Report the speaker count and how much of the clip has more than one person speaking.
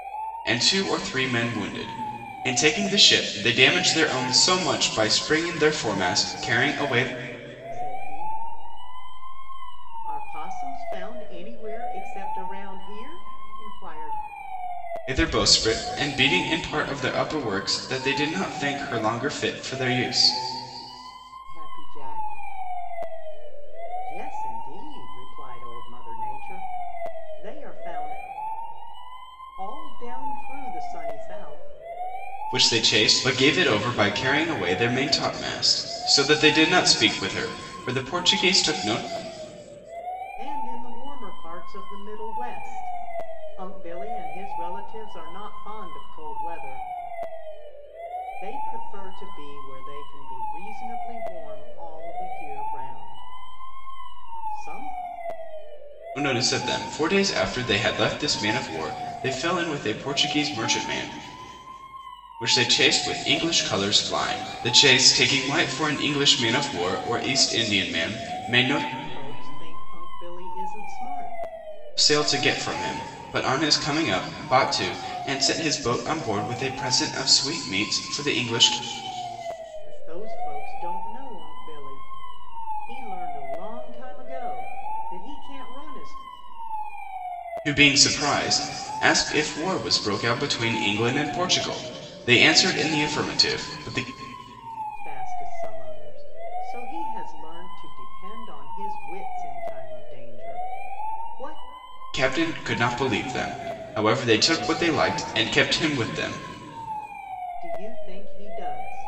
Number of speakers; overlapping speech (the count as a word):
two, no overlap